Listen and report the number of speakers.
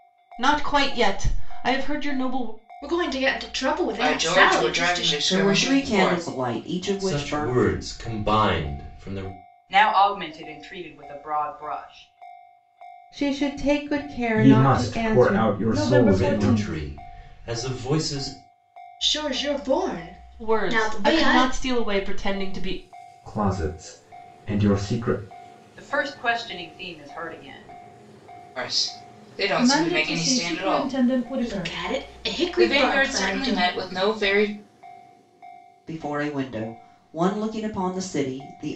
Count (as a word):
nine